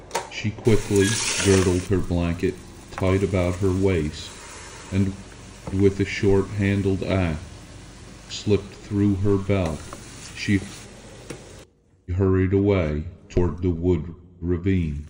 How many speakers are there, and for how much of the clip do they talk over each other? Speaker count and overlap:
1, no overlap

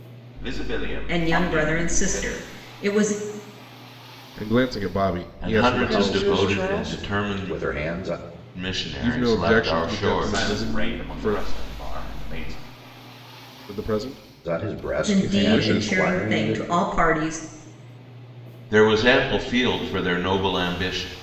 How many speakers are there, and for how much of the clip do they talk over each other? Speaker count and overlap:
5, about 38%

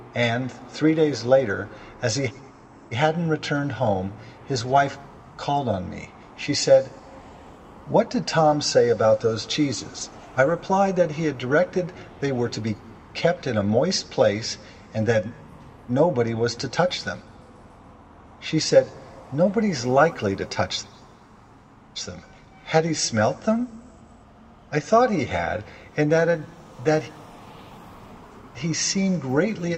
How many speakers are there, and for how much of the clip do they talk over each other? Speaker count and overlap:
1, no overlap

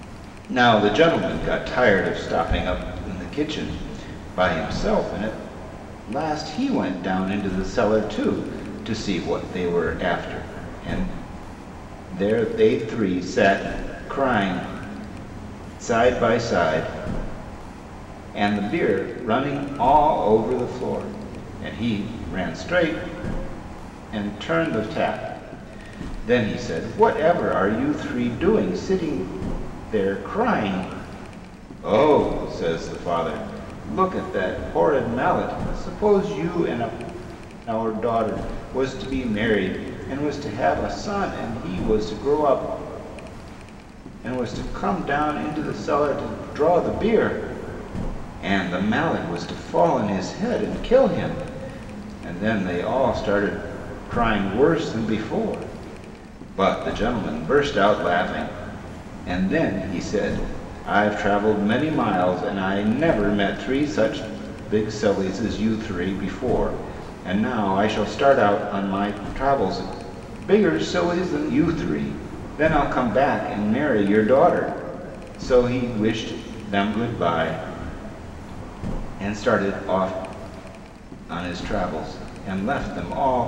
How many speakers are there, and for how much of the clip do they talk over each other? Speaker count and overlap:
1, no overlap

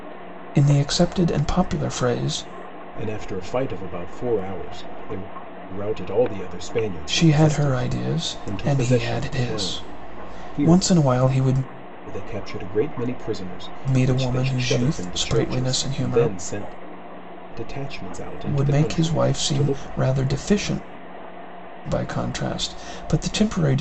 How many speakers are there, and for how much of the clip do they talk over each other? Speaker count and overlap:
2, about 30%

